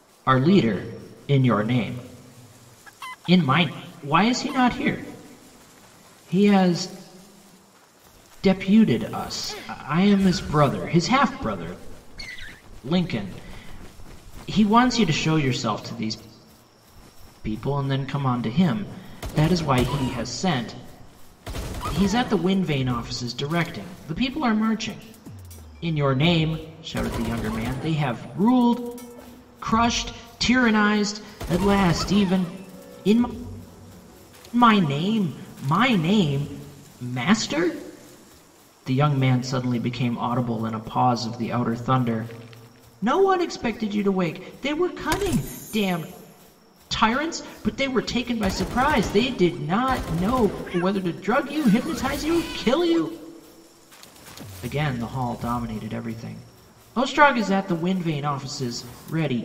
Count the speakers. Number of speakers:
1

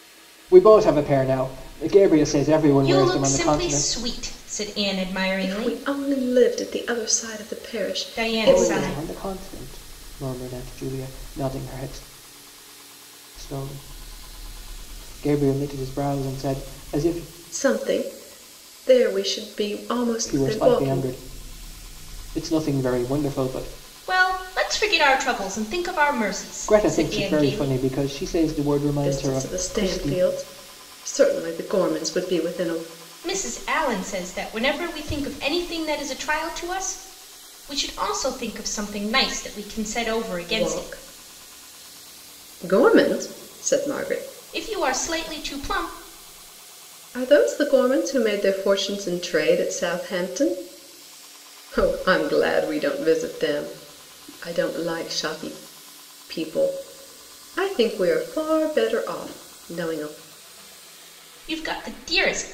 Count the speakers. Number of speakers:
3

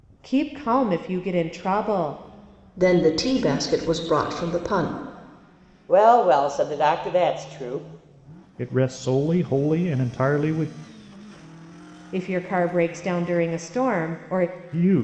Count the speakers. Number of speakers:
4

